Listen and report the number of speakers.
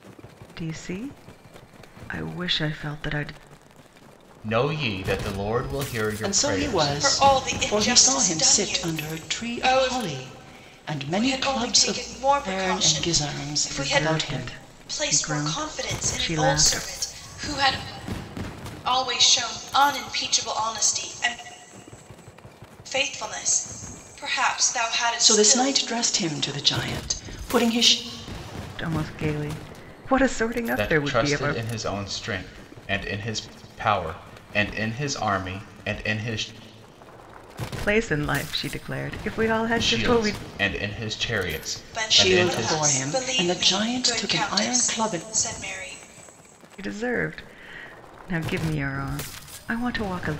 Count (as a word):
four